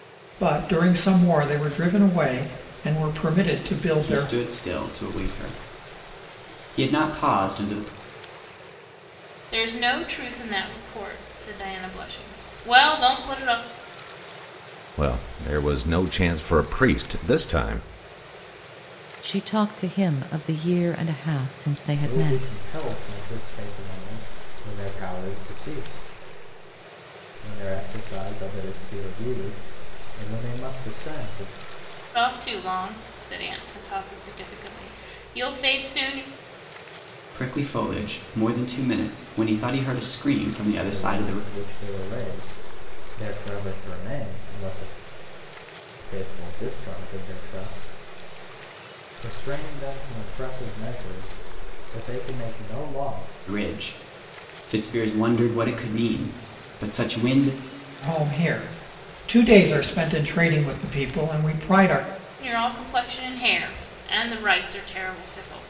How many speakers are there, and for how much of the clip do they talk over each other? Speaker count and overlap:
six, about 2%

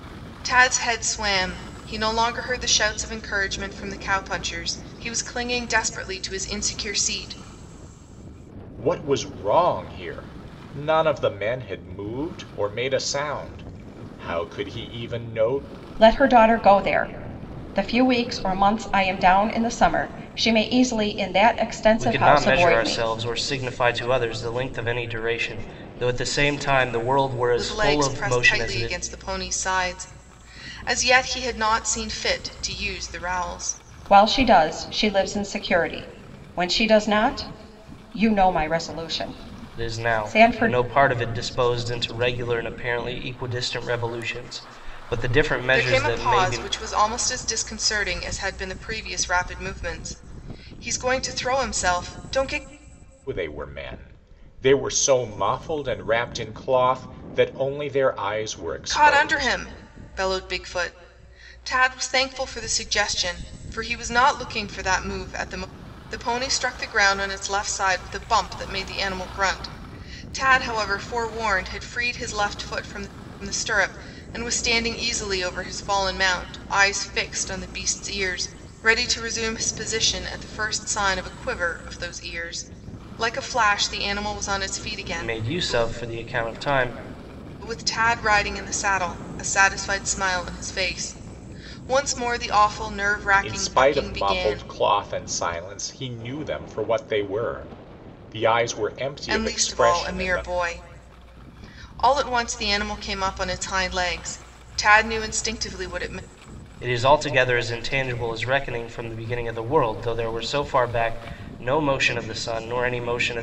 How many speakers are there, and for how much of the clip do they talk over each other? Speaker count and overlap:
four, about 8%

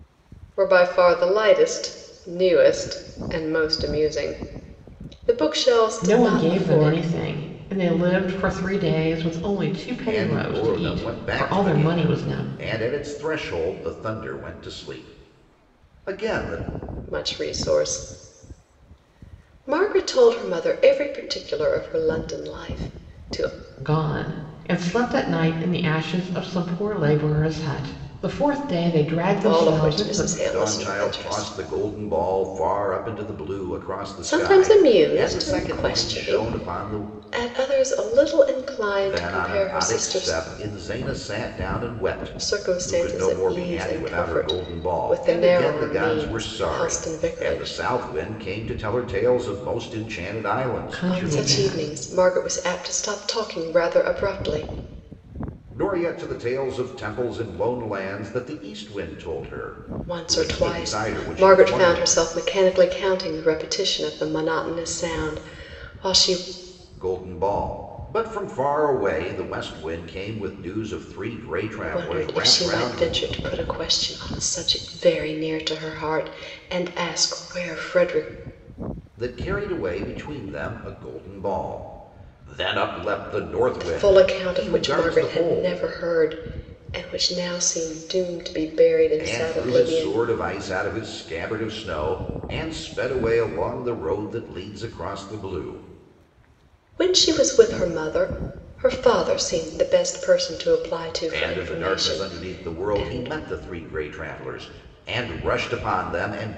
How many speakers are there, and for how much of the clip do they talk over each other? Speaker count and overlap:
three, about 23%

